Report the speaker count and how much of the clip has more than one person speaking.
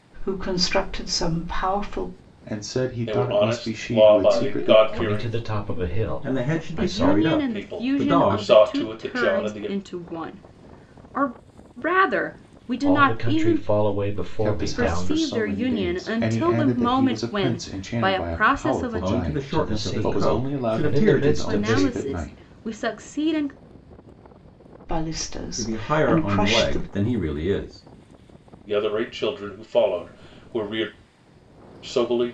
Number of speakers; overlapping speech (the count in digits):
7, about 53%